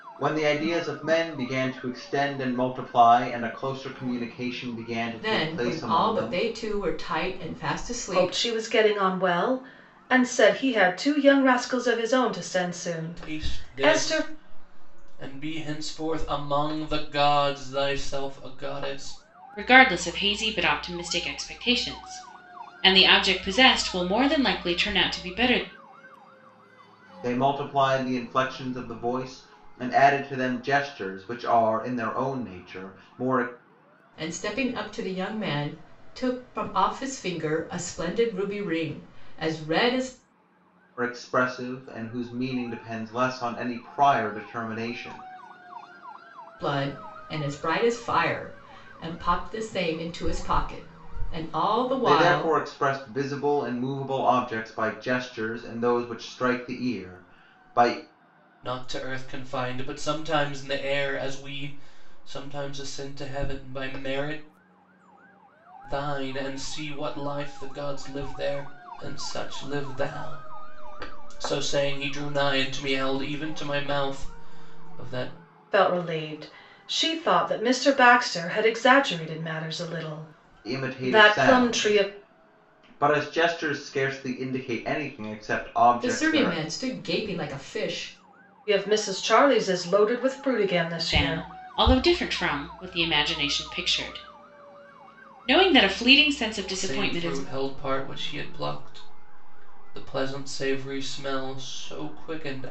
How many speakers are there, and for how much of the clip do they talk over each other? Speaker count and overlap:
5, about 6%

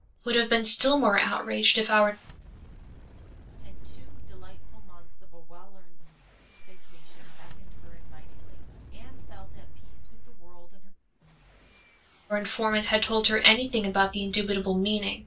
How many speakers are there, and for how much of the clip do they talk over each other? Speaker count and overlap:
2, no overlap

